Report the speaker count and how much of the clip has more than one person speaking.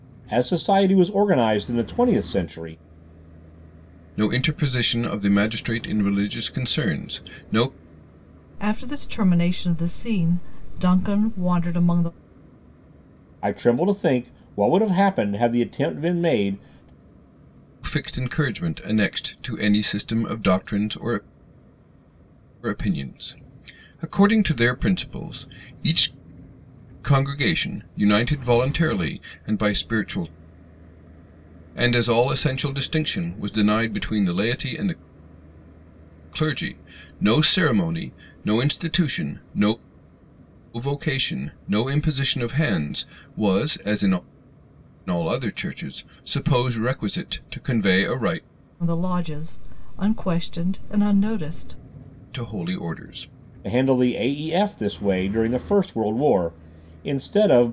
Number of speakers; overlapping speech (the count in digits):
3, no overlap